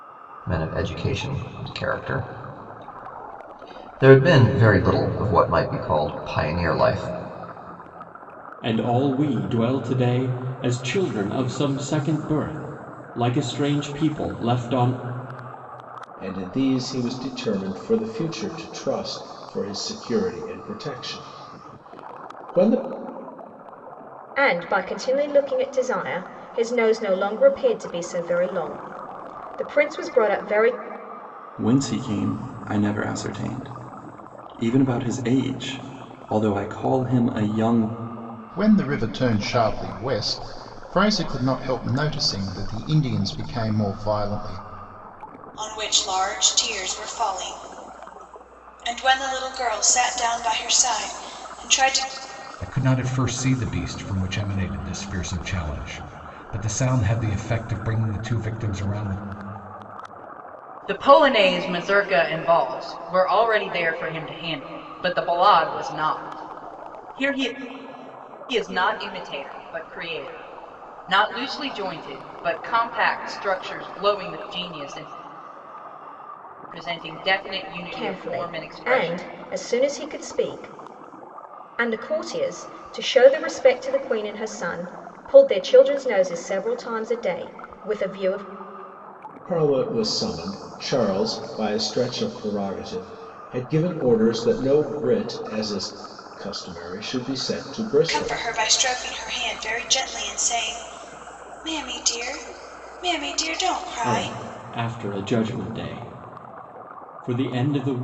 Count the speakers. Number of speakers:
nine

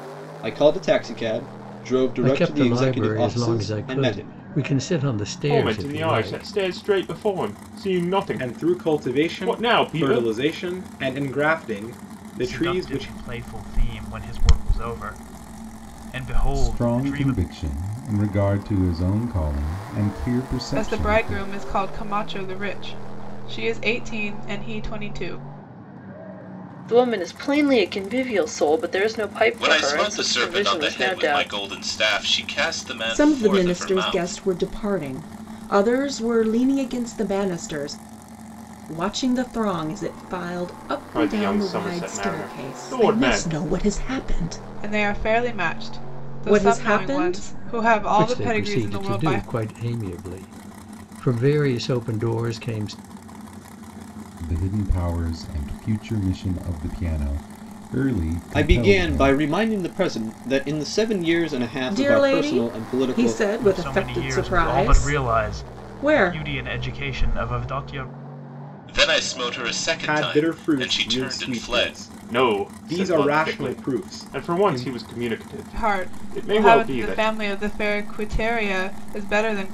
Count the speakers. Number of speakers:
ten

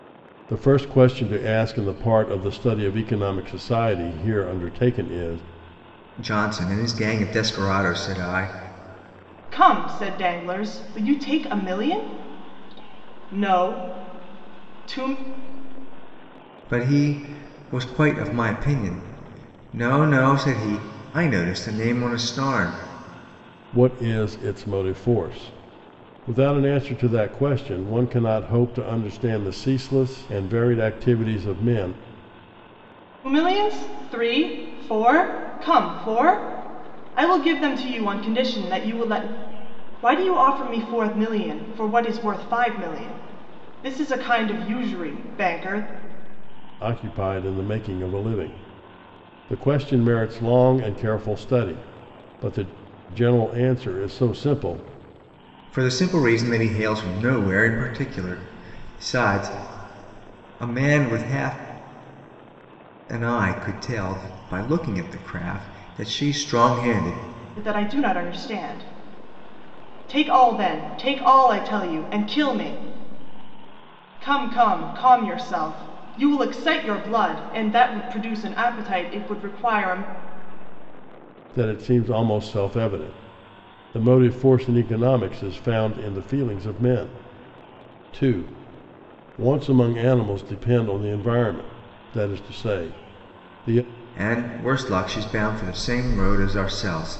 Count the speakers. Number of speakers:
three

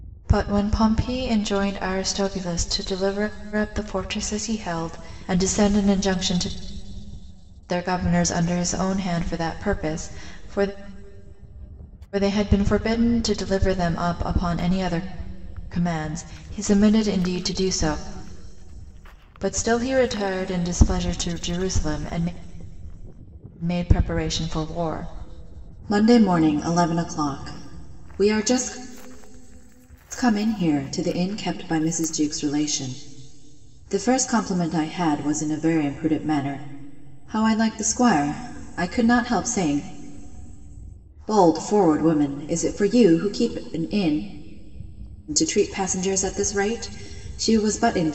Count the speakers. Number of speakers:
one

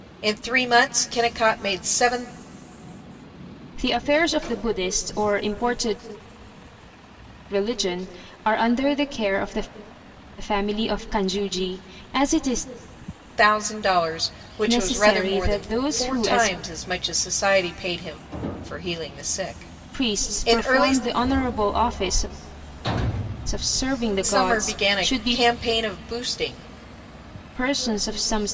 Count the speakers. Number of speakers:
two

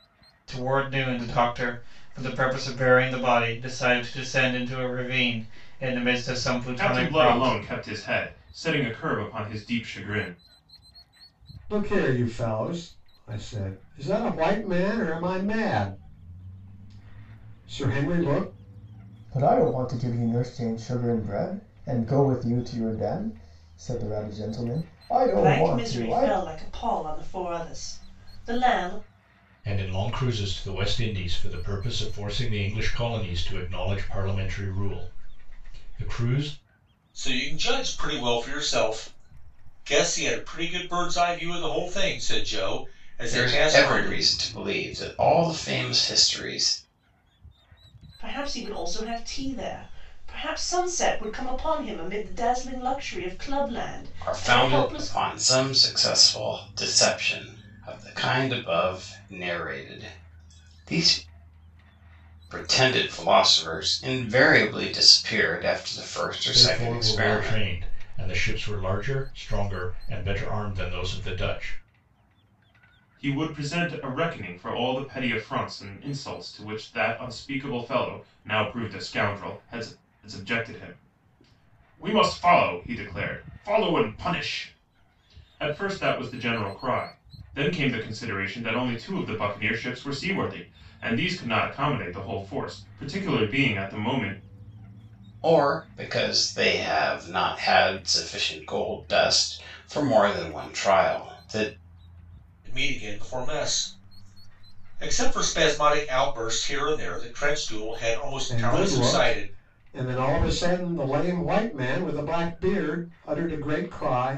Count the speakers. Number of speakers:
eight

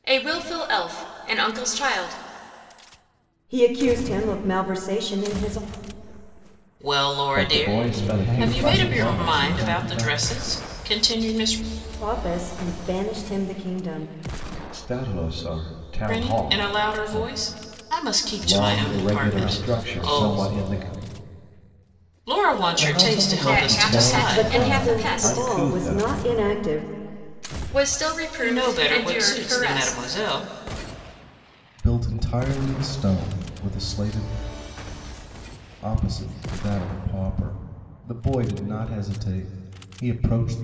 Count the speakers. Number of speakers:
five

